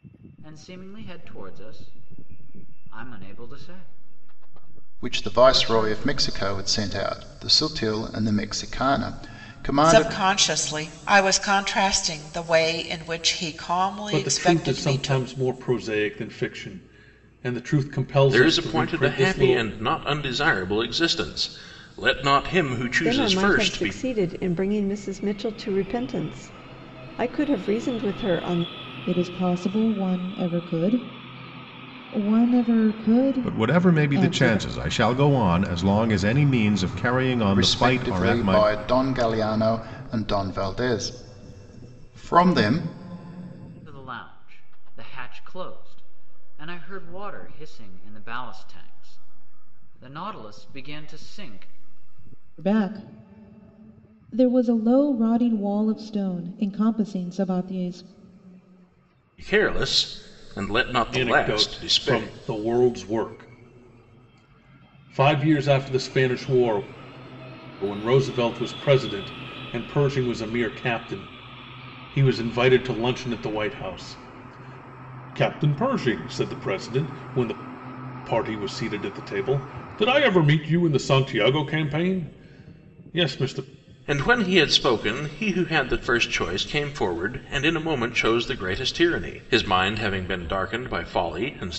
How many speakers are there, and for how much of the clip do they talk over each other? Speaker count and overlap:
8, about 10%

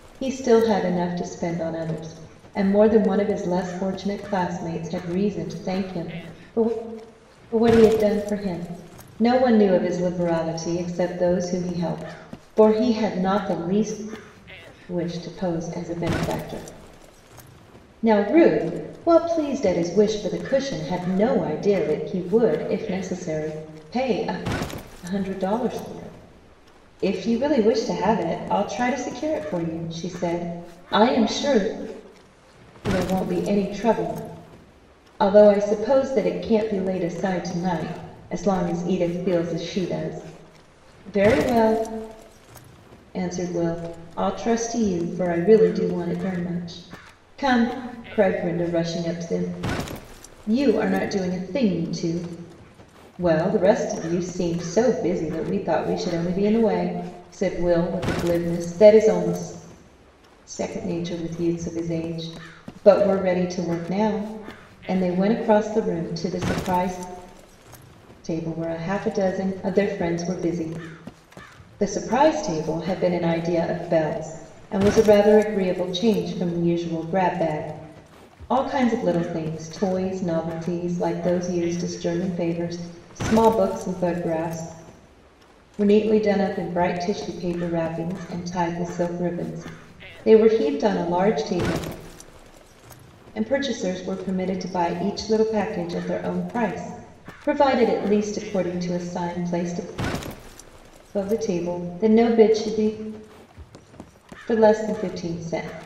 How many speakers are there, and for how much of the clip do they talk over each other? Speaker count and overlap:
1, no overlap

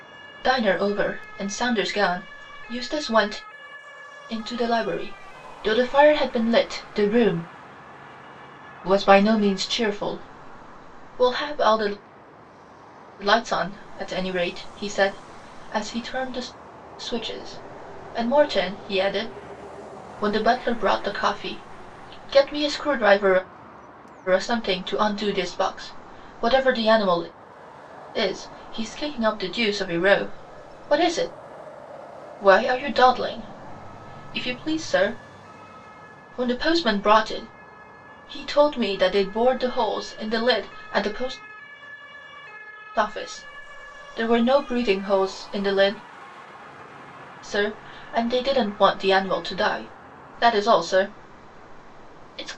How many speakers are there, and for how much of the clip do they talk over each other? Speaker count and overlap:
1, no overlap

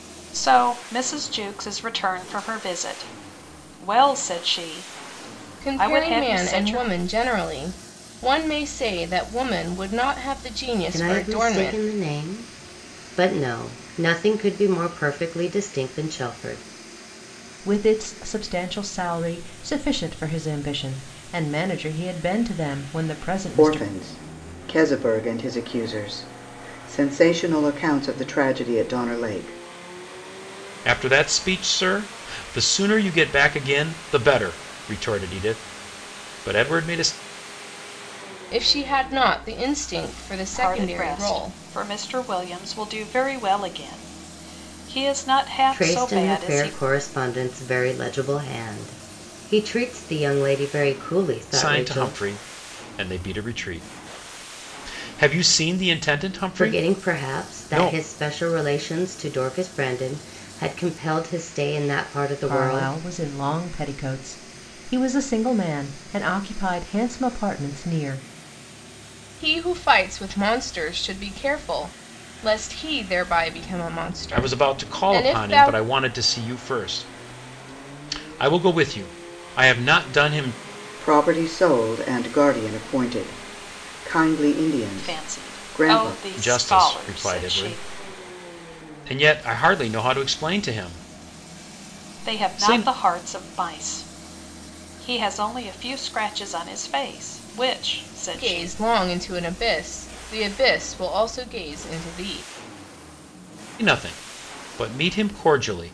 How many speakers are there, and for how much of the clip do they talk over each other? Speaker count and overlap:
6, about 12%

